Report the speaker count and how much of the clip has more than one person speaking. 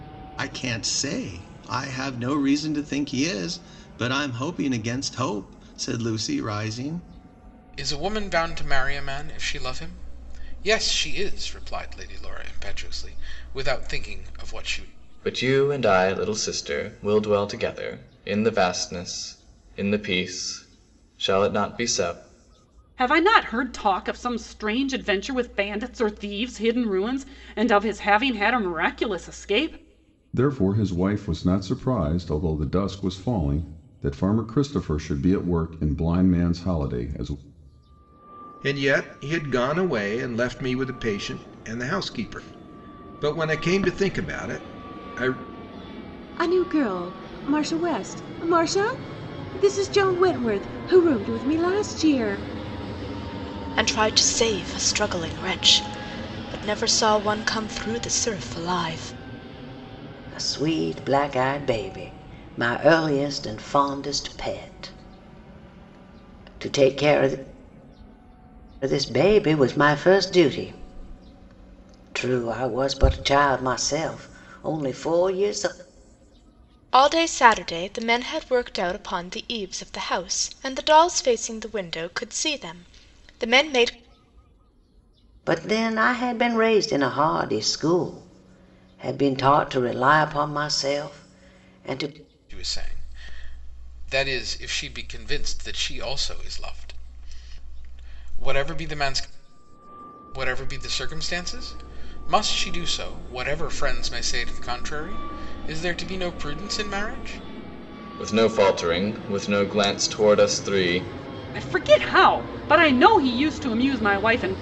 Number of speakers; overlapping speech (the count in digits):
9, no overlap